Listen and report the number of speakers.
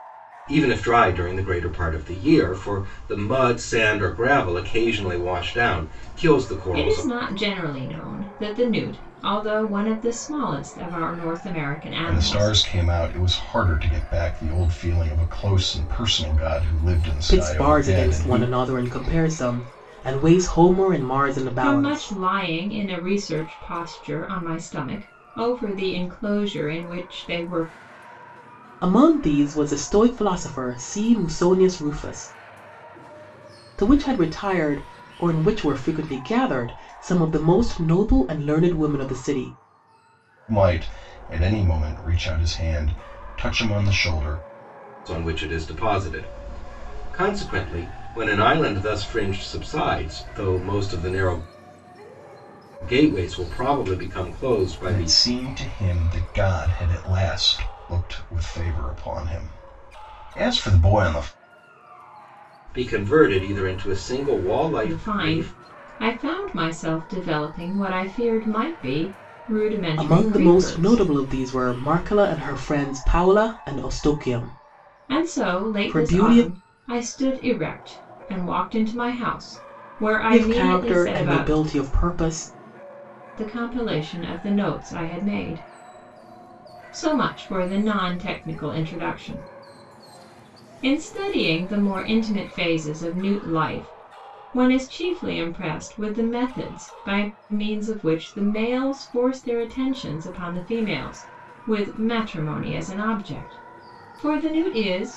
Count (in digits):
4